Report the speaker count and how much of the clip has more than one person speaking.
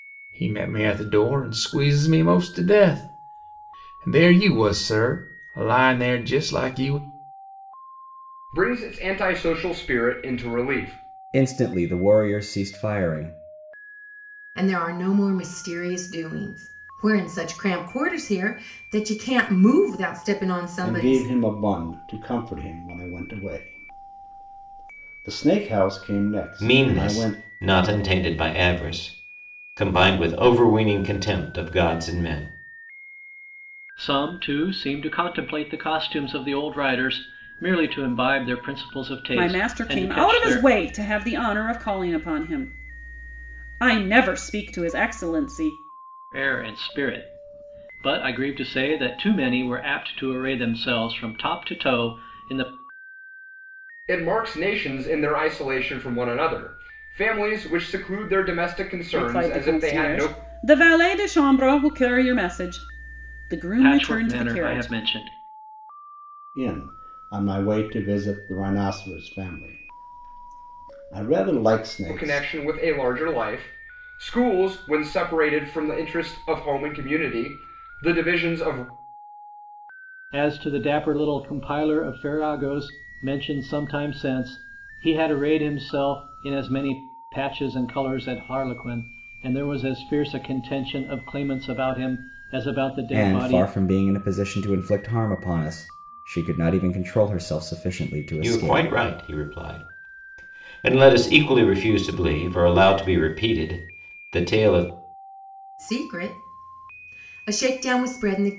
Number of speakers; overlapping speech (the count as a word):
eight, about 6%